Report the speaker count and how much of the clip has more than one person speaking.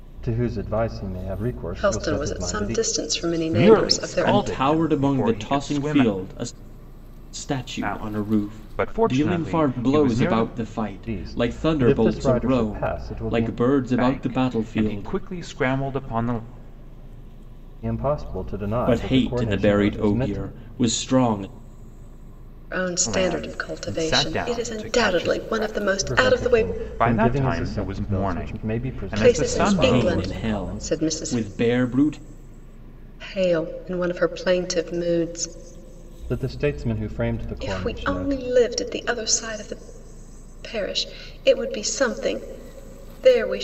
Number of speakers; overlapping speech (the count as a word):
four, about 48%